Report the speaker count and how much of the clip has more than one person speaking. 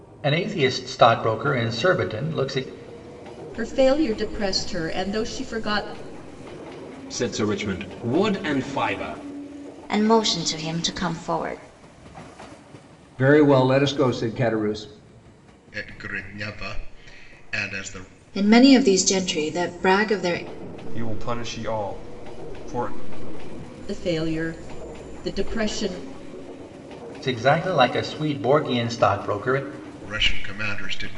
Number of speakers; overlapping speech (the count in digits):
8, no overlap